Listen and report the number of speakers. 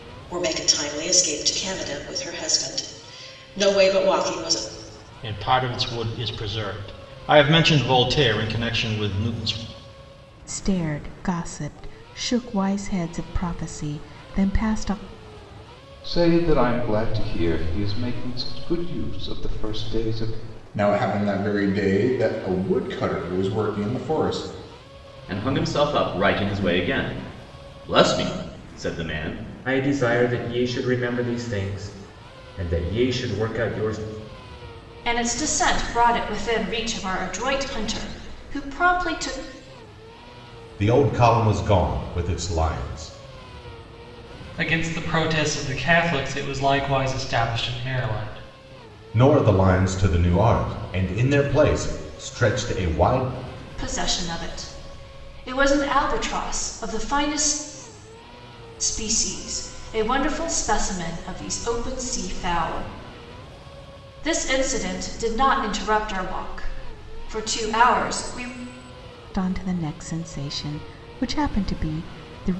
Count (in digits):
10